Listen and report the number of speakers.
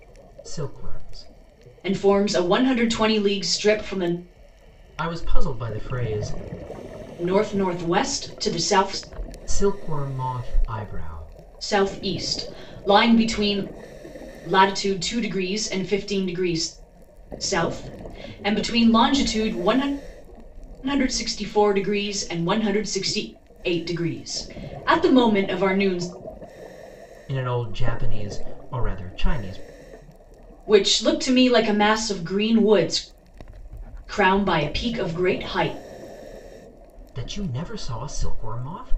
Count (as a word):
two